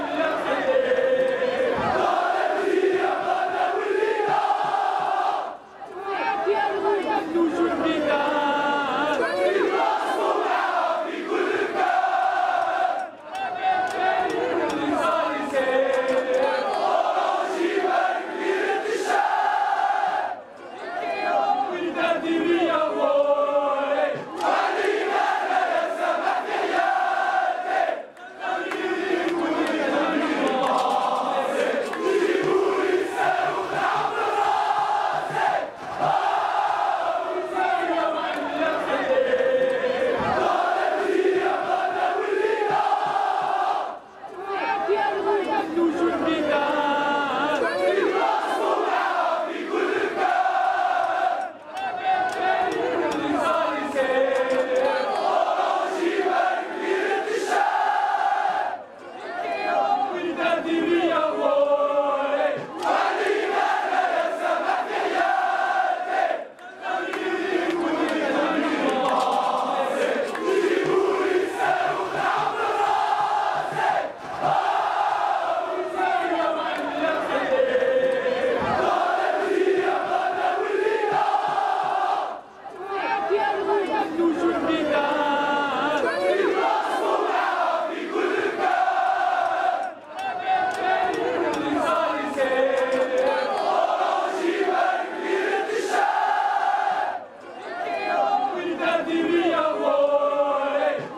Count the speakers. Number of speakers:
0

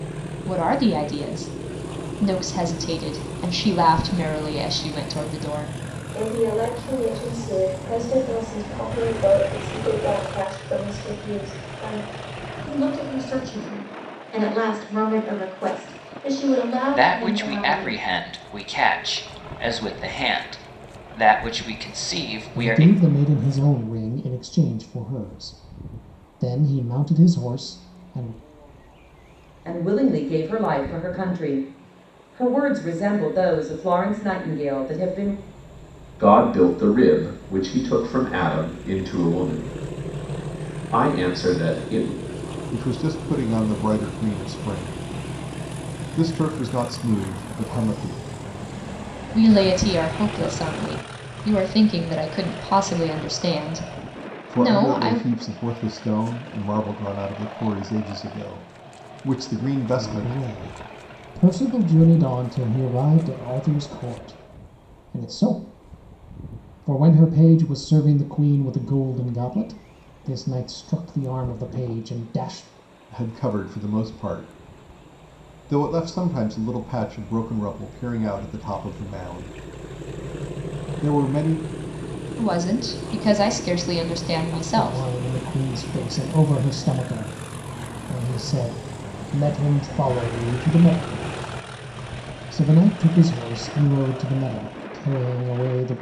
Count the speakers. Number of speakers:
8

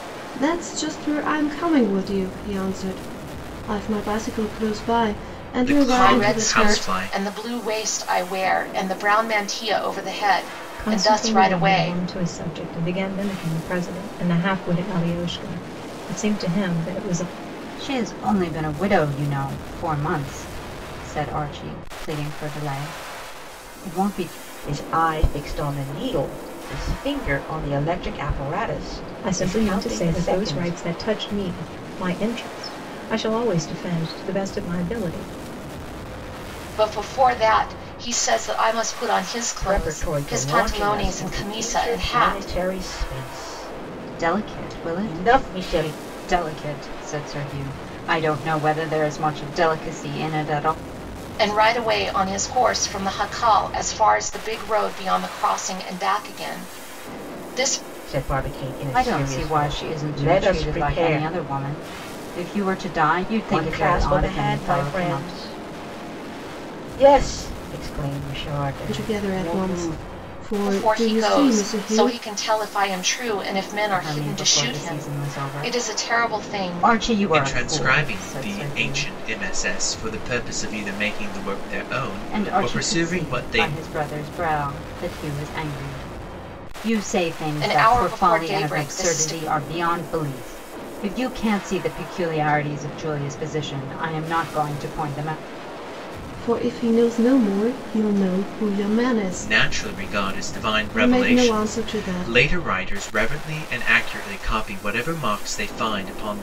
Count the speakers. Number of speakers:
6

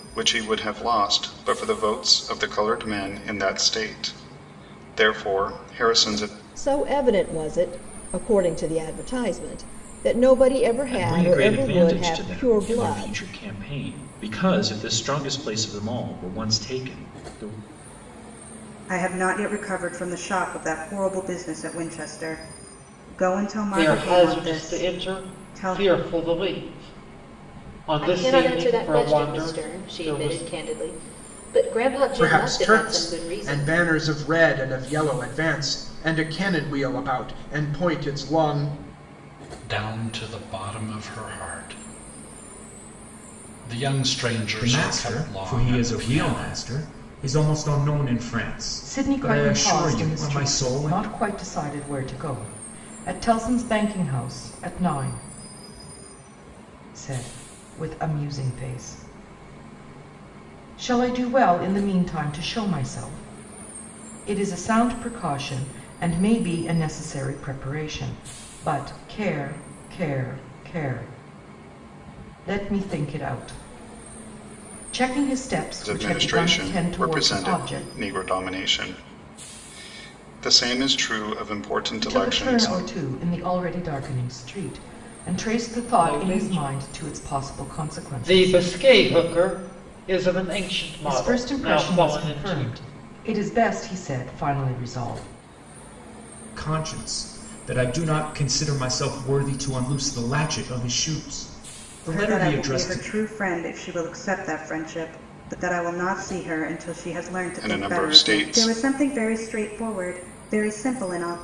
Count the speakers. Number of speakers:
10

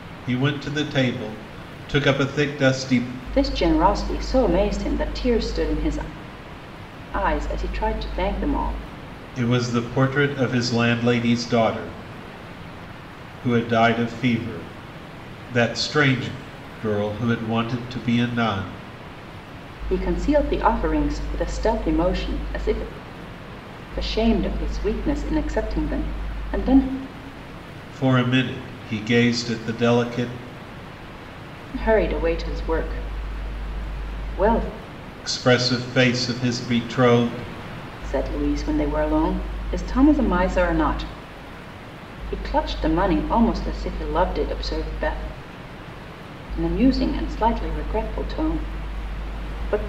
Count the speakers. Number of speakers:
2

